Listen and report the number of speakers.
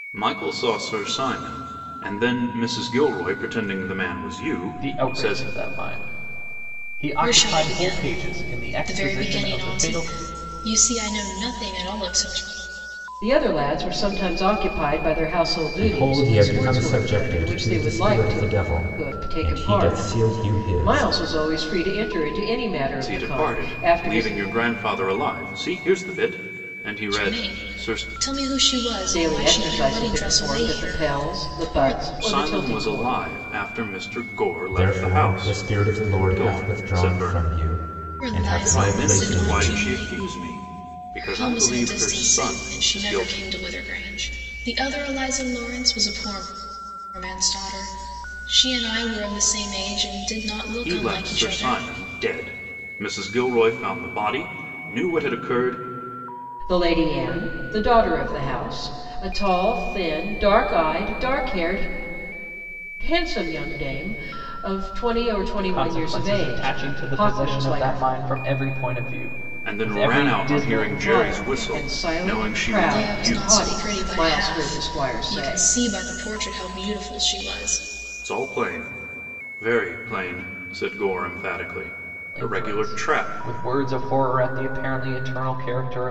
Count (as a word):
five